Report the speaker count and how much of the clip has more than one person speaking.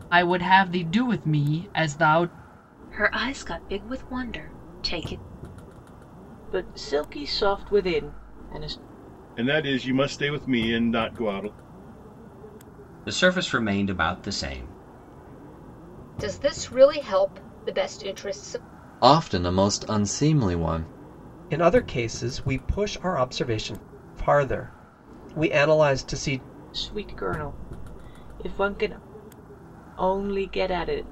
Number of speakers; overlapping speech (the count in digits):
8, no overlap